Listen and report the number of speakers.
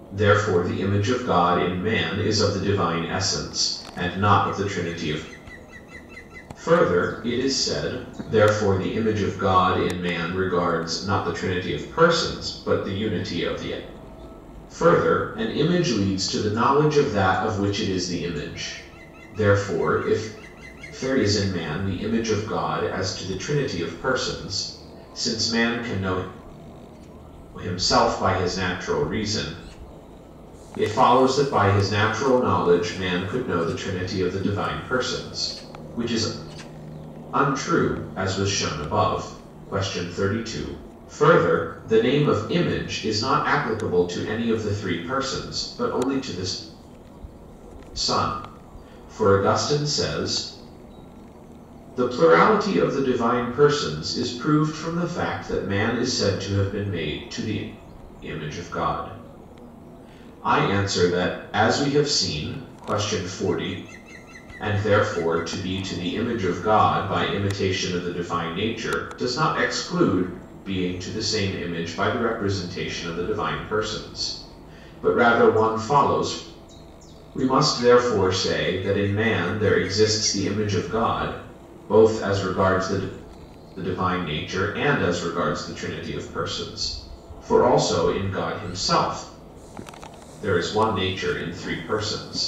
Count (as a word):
one